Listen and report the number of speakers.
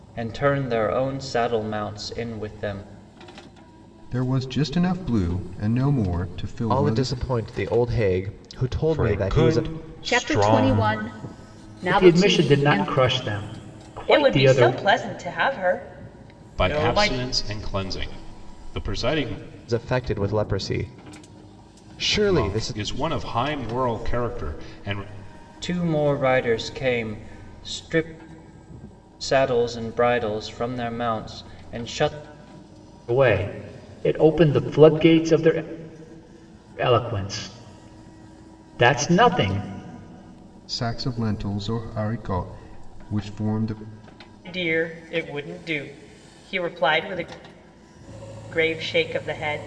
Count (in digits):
8